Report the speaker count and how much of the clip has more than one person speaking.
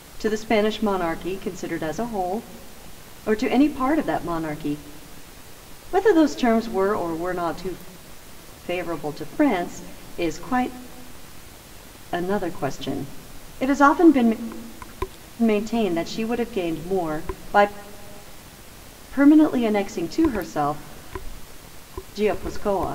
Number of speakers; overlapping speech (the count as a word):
one, no overlap